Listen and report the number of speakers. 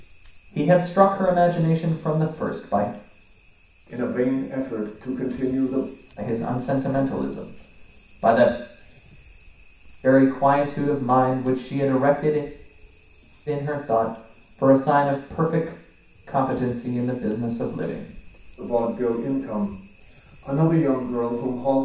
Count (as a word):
two